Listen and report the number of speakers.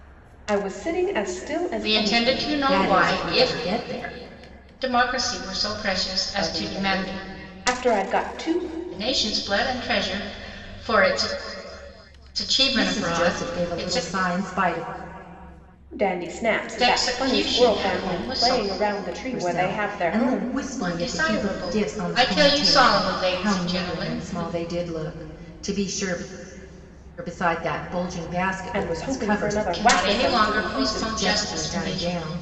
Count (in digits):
3